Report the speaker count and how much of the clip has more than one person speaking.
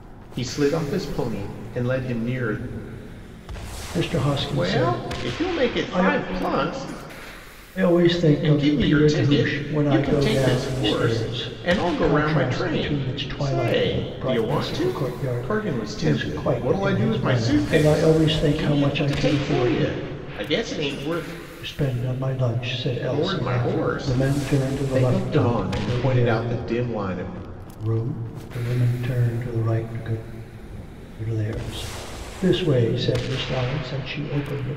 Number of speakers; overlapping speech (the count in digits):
2, about 43%